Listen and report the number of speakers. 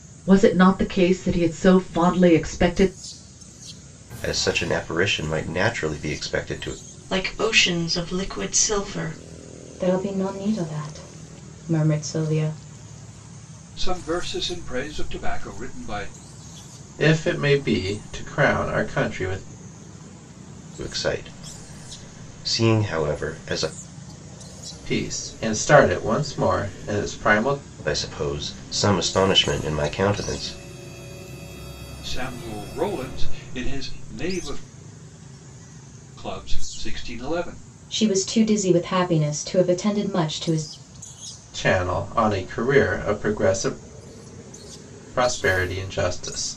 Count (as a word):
six